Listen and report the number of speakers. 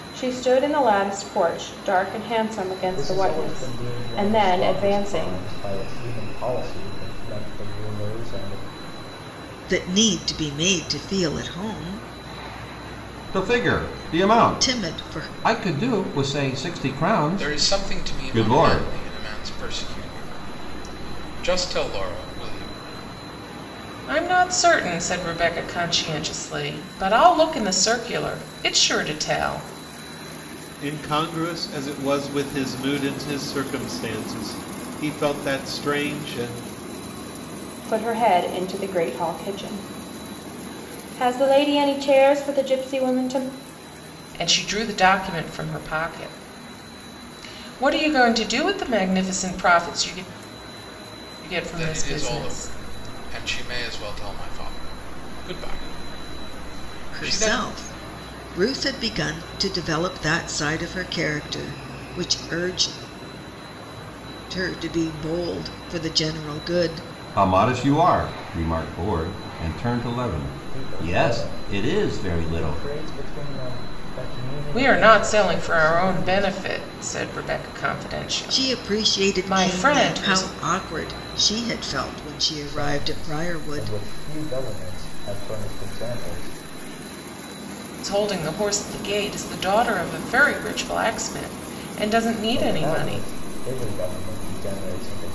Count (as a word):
seven